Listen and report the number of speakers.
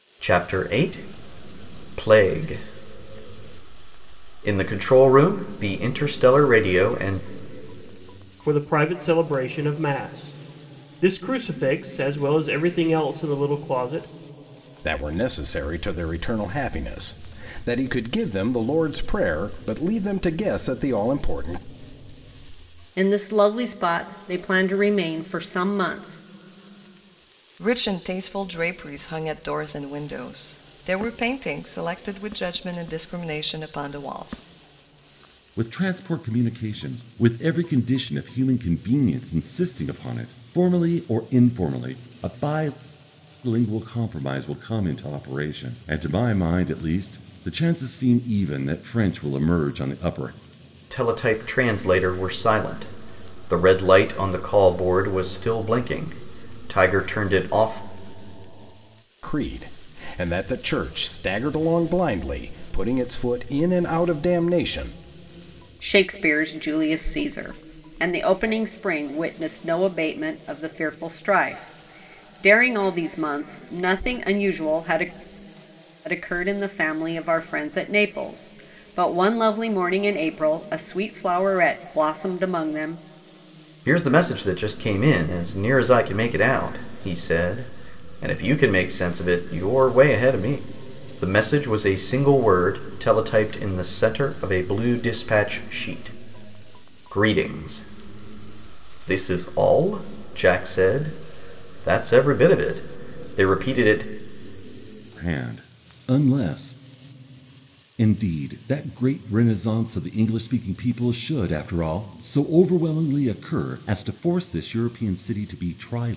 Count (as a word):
six